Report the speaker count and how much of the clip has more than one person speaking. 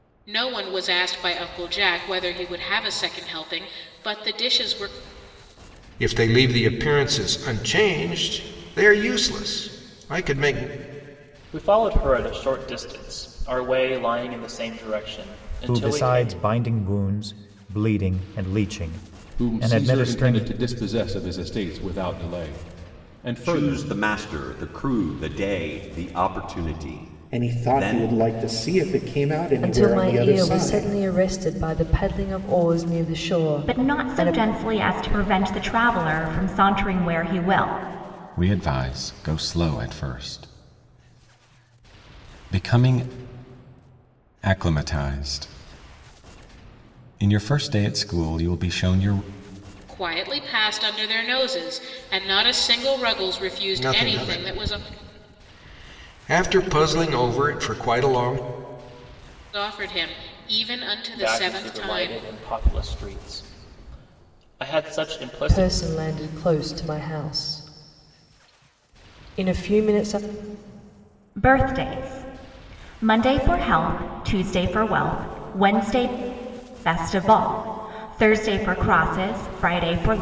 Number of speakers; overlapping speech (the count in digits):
10, about 10%